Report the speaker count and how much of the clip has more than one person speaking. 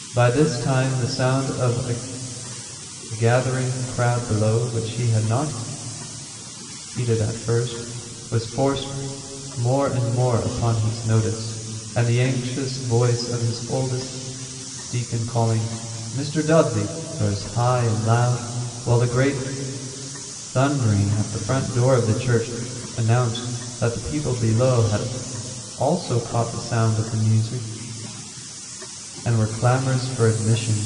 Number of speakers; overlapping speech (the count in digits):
1, no overlap